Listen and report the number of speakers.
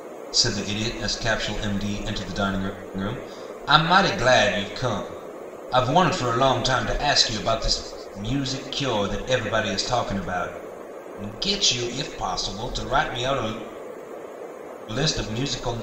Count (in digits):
1